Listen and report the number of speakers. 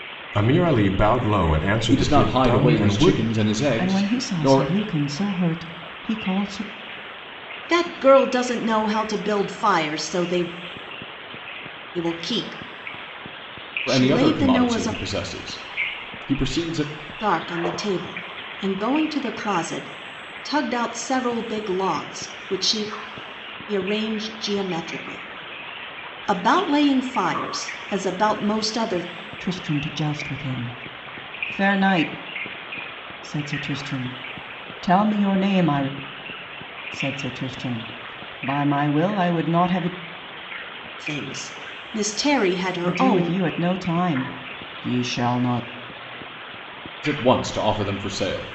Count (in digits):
4